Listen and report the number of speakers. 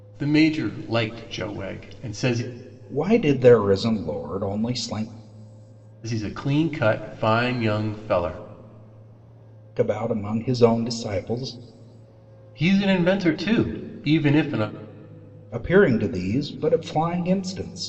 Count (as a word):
two